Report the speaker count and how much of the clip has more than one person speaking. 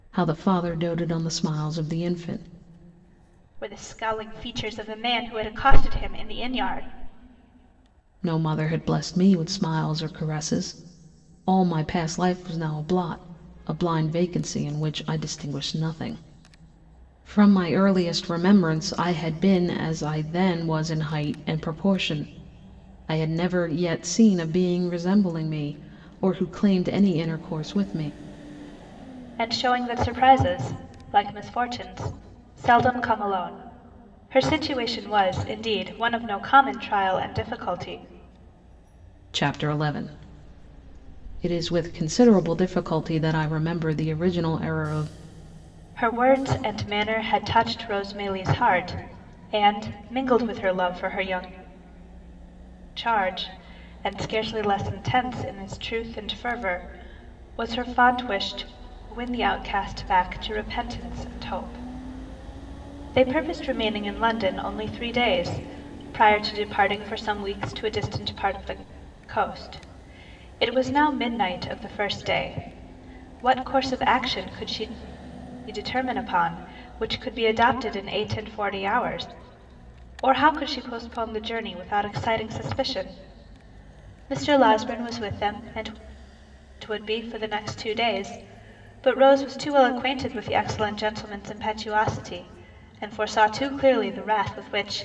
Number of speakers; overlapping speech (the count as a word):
two, no overlap